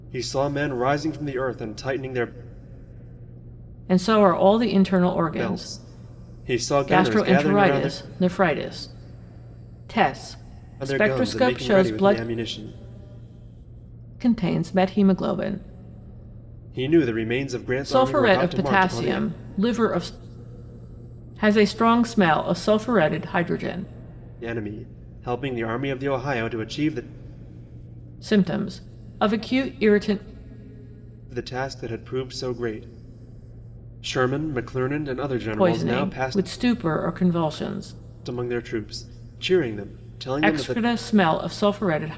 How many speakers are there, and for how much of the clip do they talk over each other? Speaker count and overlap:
2, about 14%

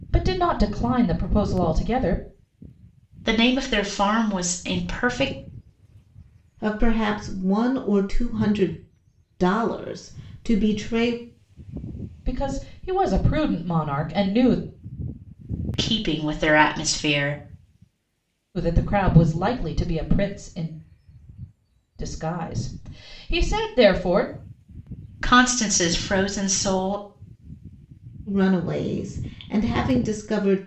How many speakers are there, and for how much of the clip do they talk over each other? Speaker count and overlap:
3, no overlap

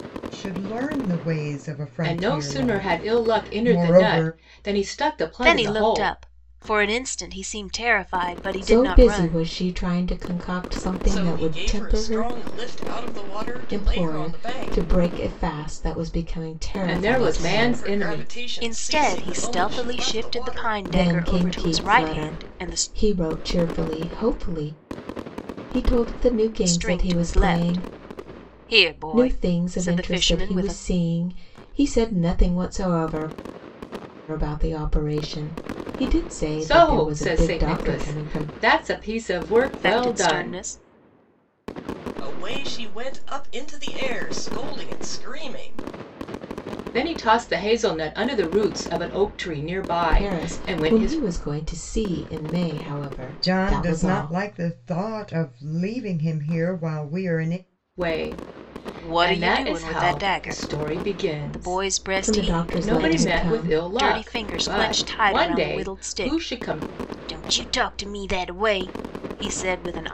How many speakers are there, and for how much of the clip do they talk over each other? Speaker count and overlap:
5, about 39%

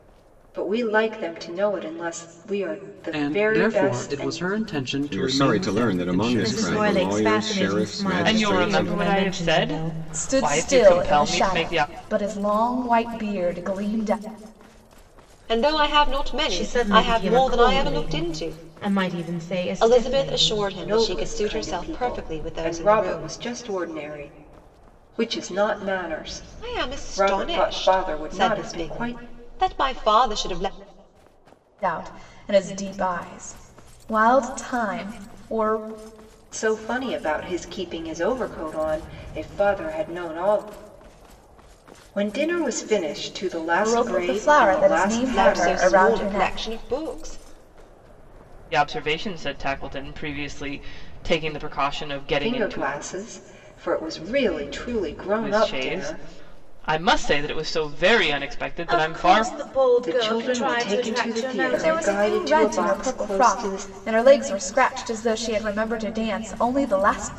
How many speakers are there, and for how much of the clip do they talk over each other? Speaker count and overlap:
7, about 37%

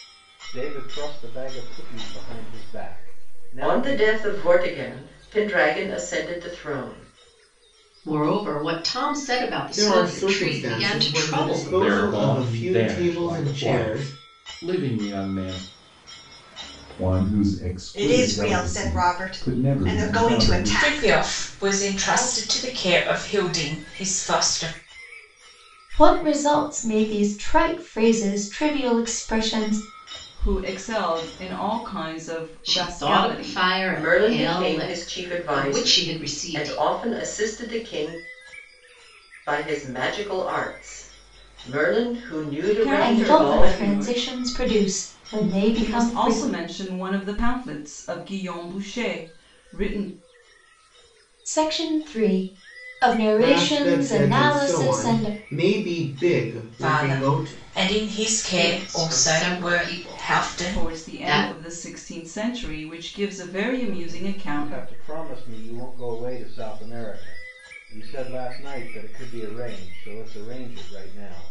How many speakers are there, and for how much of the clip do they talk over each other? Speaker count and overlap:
10, about 33%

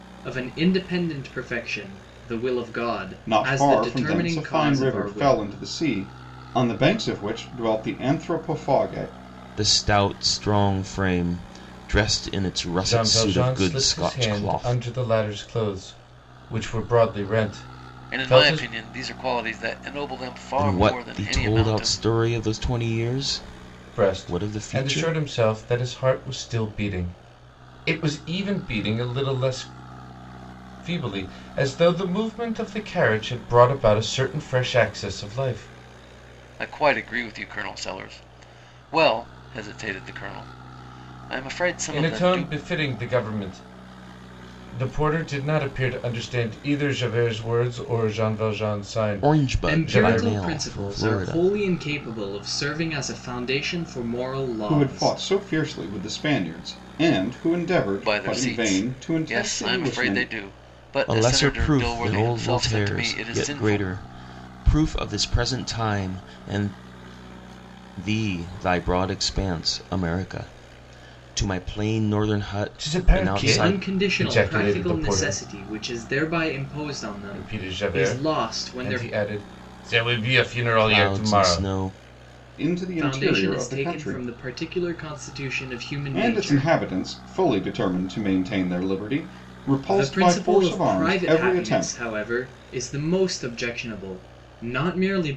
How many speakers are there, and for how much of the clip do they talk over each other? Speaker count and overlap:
5, about 27%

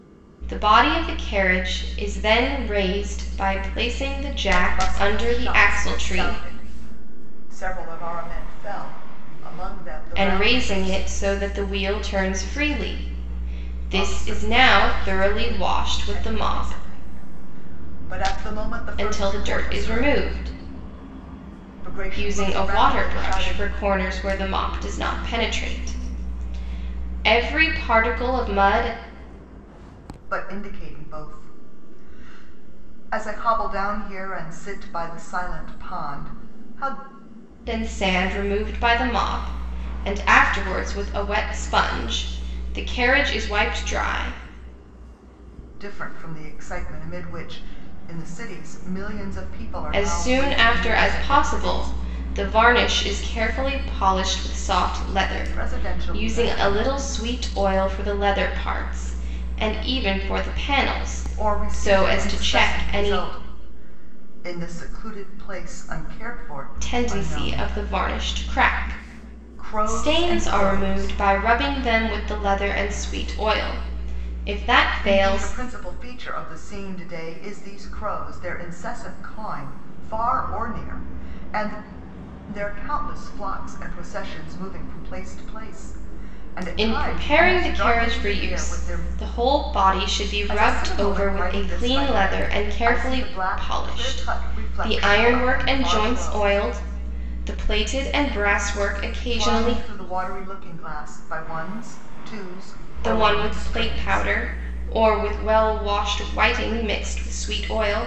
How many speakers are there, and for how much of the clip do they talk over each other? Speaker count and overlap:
2, about 25%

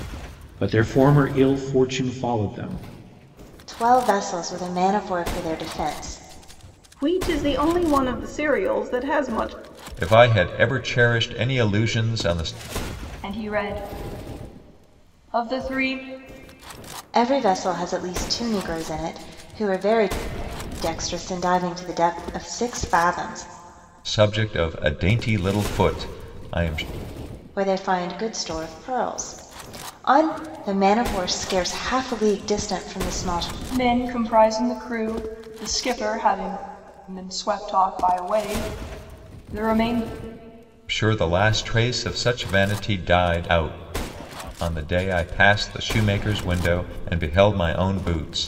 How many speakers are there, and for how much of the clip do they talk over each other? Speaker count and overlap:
5, no overlap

